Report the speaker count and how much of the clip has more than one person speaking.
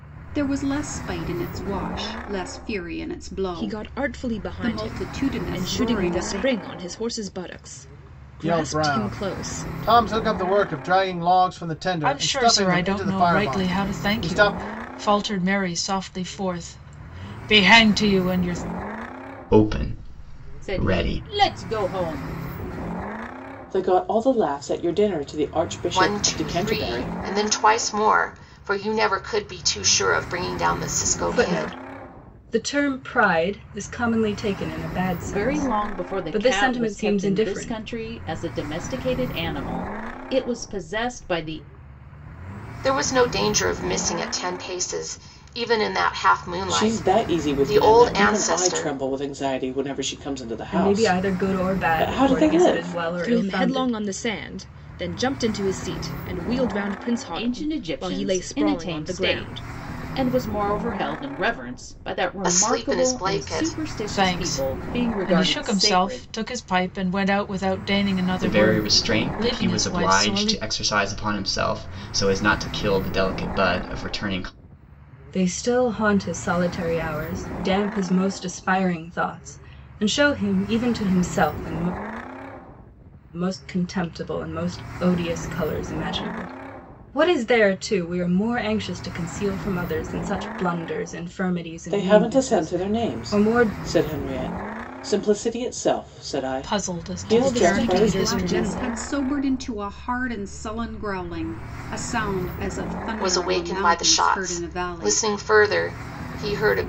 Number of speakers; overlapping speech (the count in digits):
9, about 30%